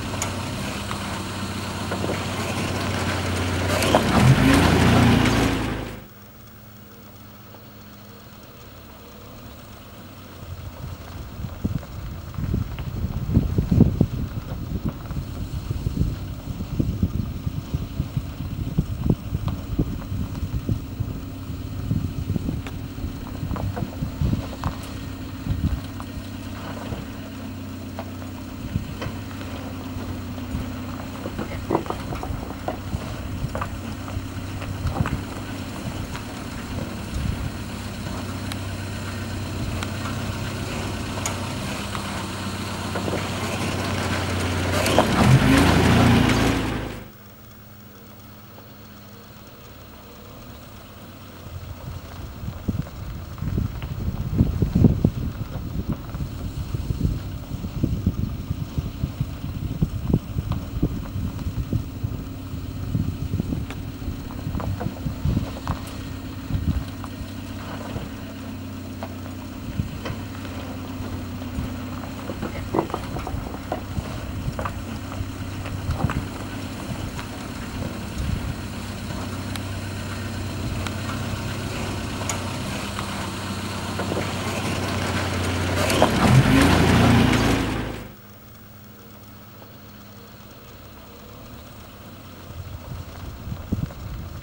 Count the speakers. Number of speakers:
zero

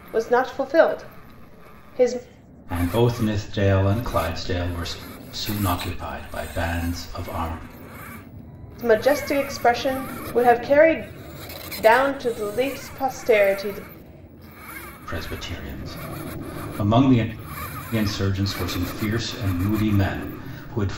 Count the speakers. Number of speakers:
two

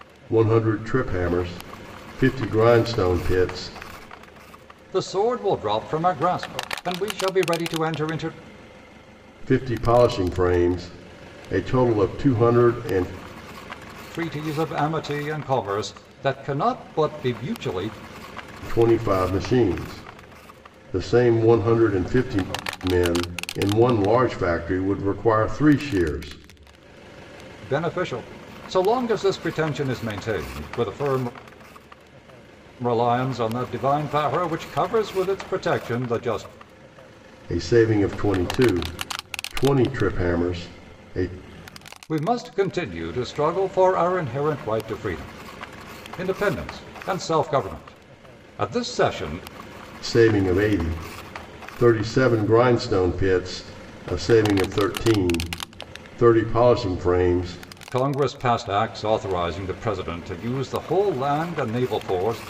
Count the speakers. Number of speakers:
two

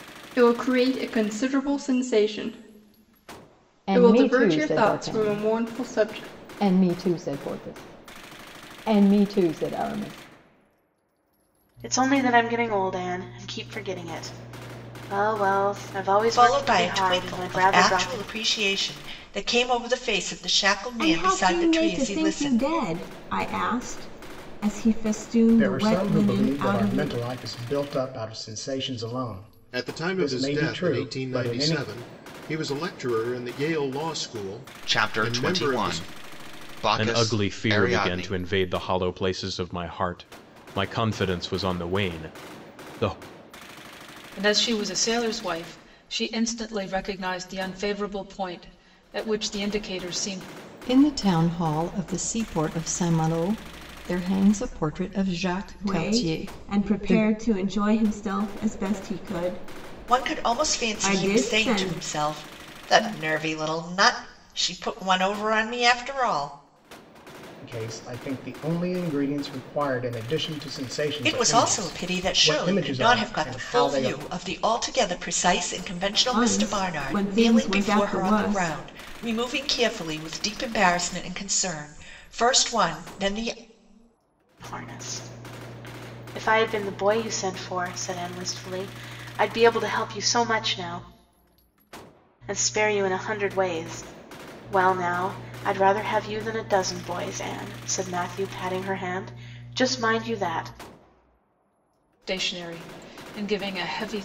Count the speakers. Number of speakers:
ten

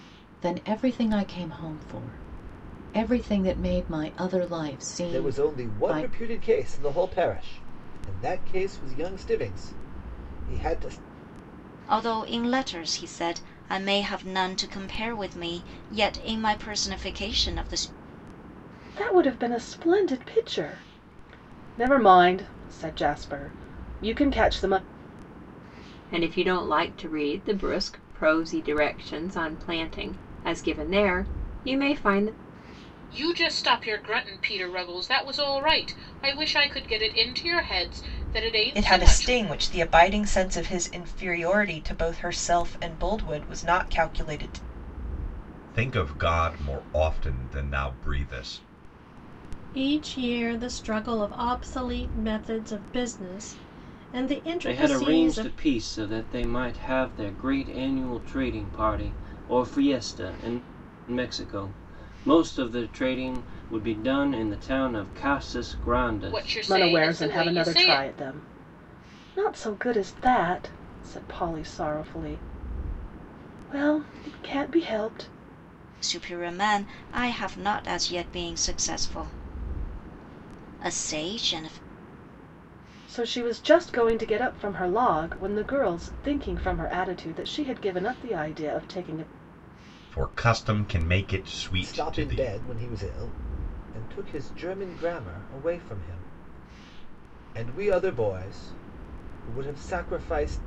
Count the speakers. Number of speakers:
ten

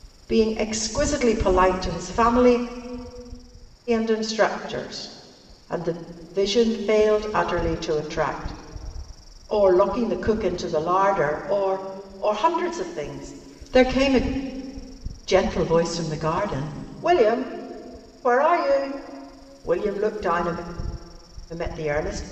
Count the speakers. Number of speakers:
one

